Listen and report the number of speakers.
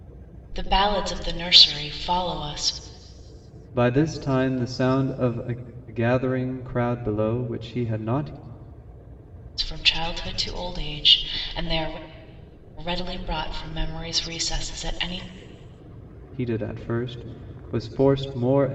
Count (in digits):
2